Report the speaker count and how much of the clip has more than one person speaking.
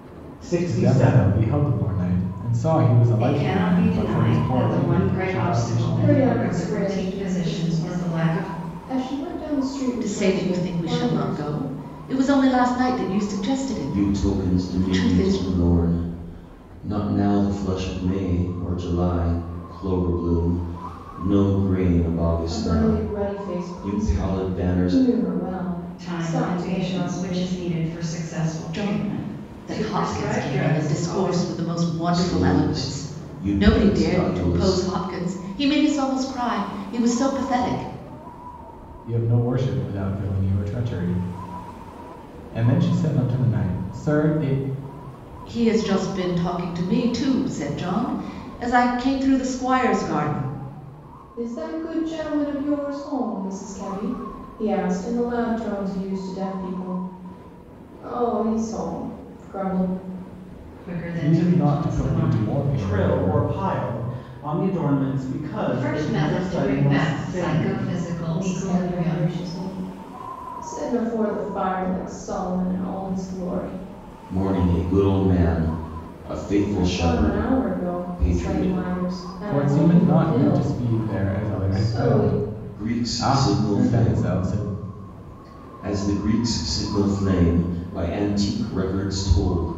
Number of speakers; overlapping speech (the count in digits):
6, about 35%